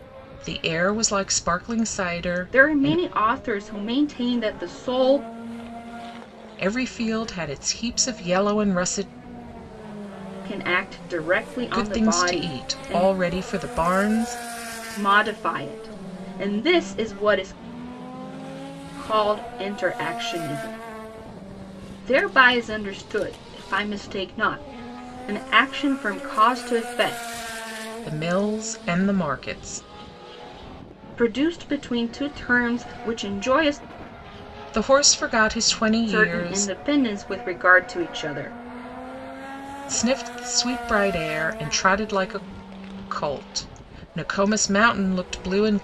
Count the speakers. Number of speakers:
two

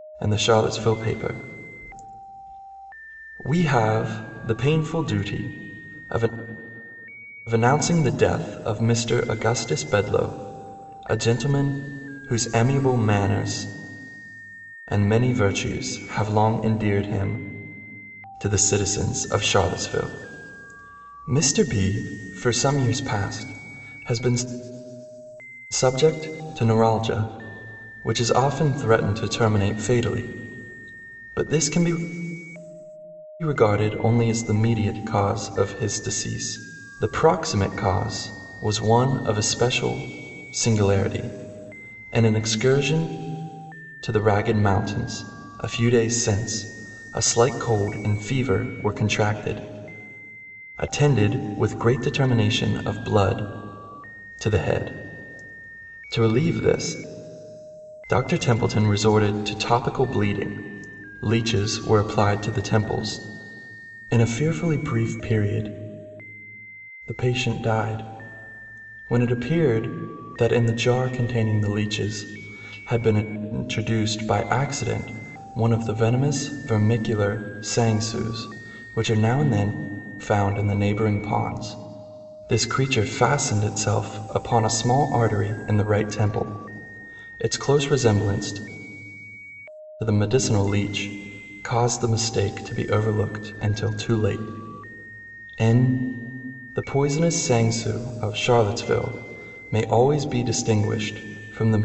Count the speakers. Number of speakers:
one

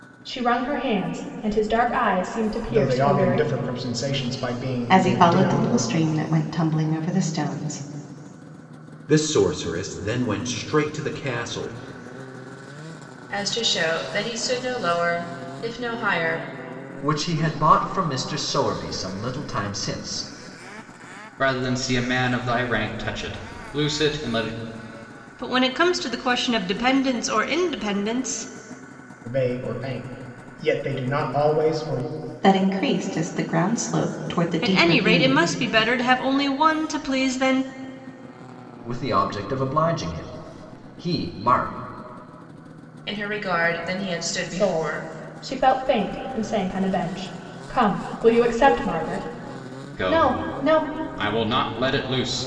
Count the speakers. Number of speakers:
eight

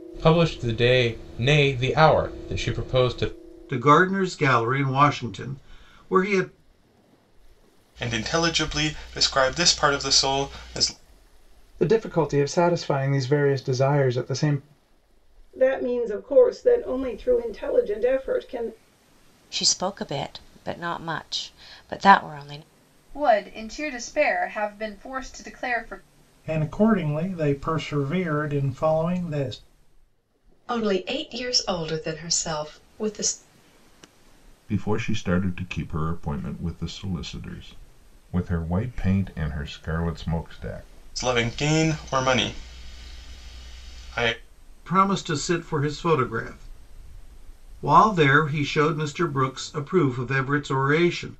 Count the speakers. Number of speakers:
ten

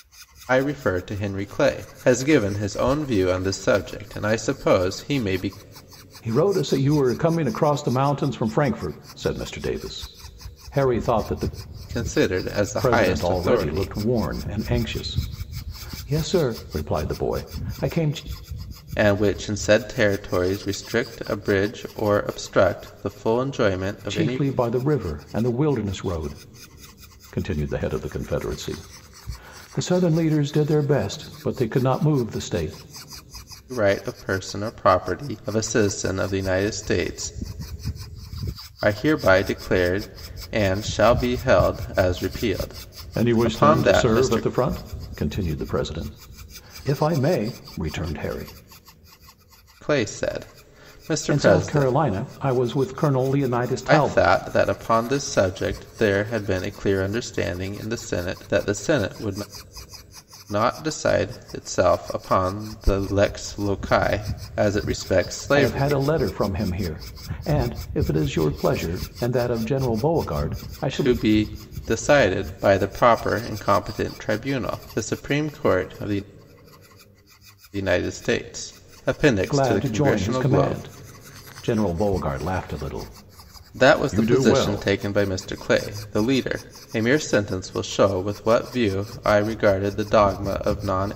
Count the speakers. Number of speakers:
two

